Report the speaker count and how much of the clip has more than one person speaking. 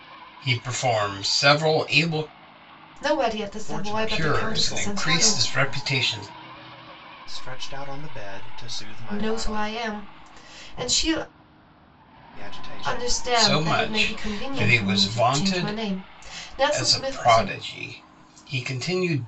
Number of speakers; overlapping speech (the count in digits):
3, about 34%